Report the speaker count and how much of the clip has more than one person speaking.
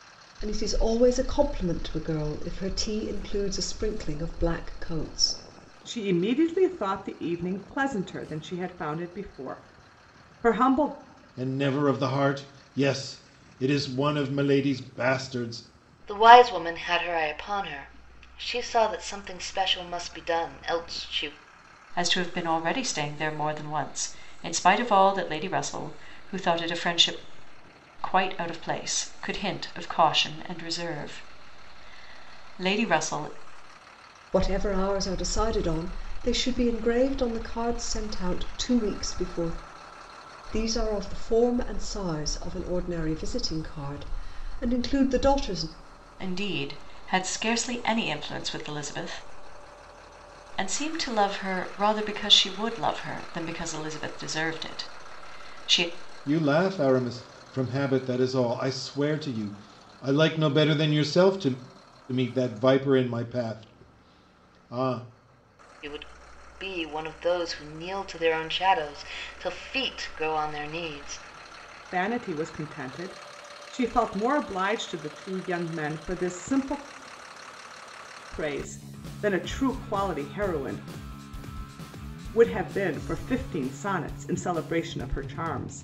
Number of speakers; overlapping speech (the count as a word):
five, no overlap